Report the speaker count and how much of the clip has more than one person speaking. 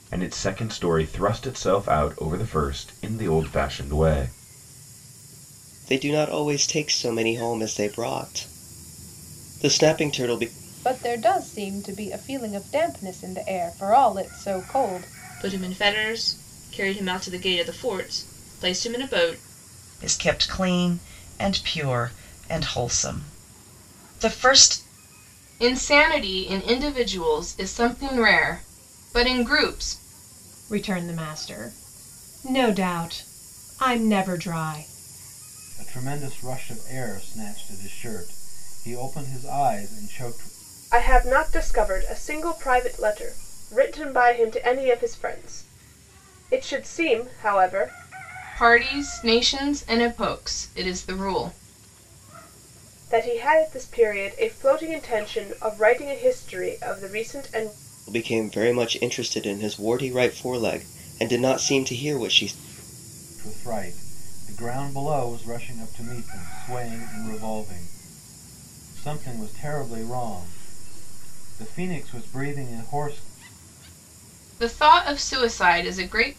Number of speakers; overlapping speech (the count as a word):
nine, no overlap